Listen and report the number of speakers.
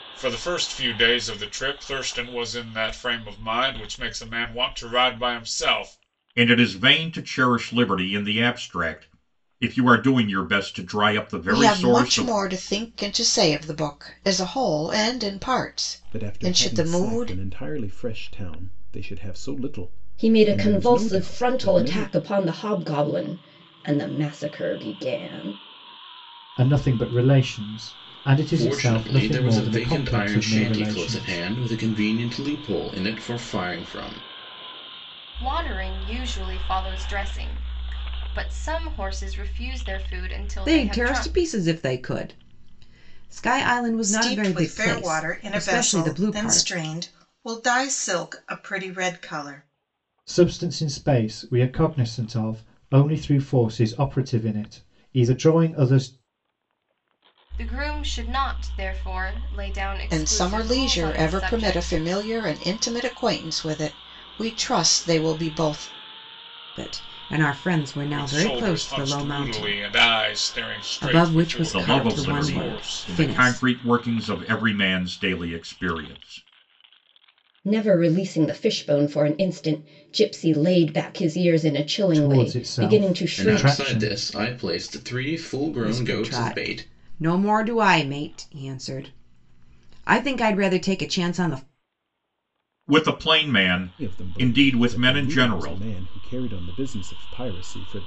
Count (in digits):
10